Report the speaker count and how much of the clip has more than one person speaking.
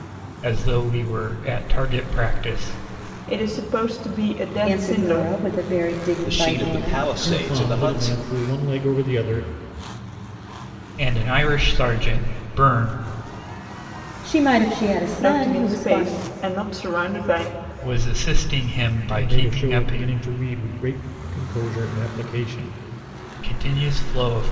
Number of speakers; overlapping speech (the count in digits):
5, about 20%